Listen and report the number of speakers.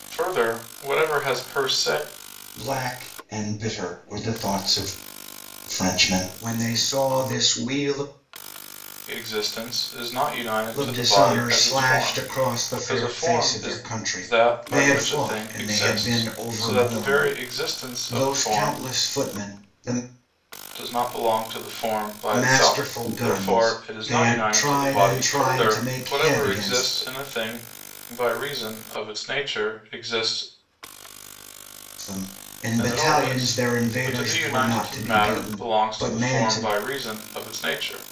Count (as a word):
two